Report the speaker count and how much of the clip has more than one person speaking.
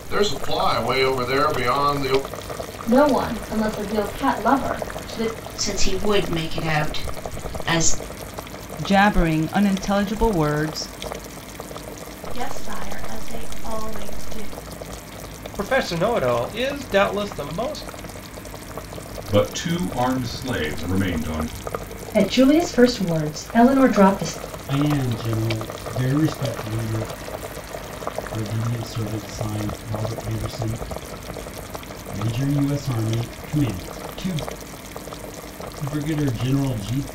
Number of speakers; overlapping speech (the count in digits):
9, no overlap